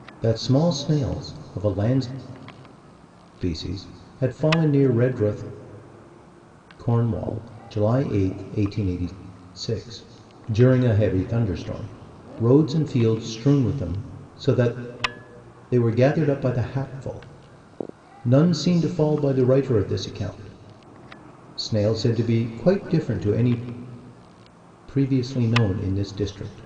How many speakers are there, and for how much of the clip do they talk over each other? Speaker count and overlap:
1, no overlap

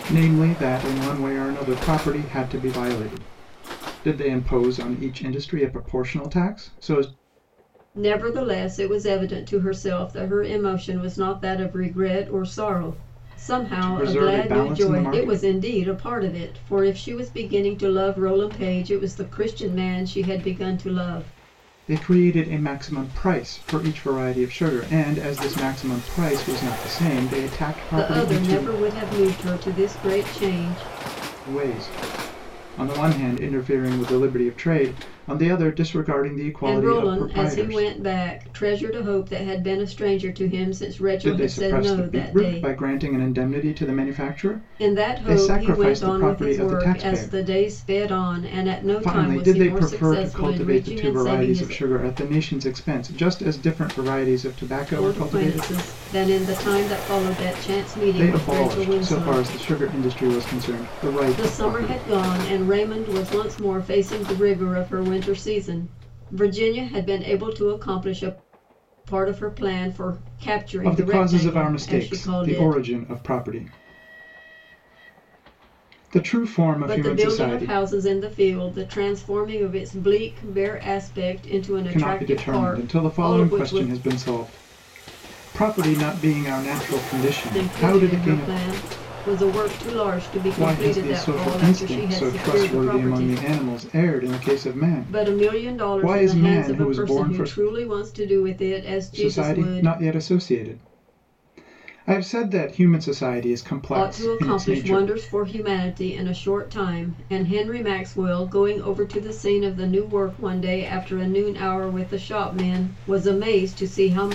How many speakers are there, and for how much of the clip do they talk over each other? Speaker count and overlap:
2, about 24%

